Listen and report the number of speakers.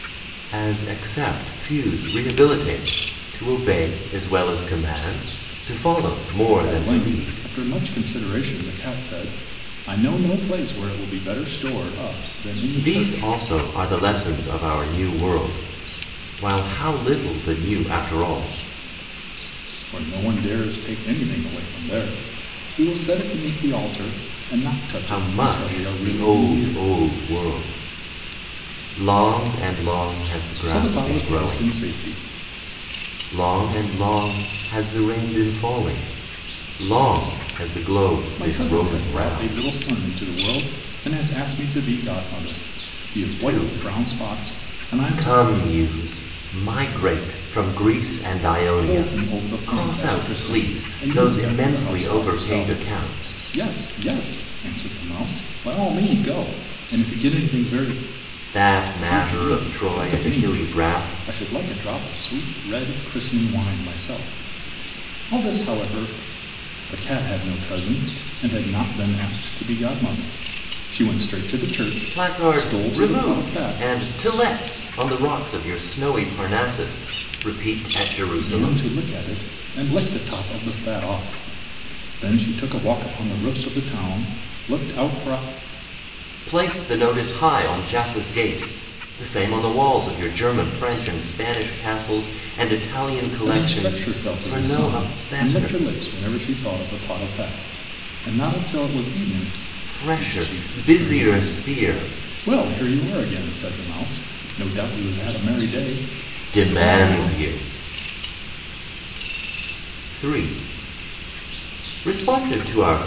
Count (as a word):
two